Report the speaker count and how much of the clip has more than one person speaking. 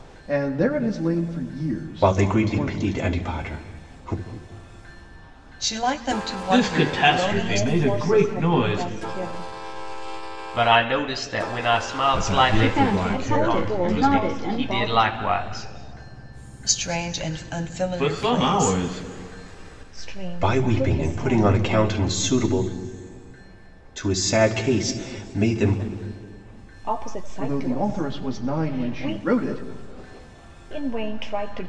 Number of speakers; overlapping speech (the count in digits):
8, about 34%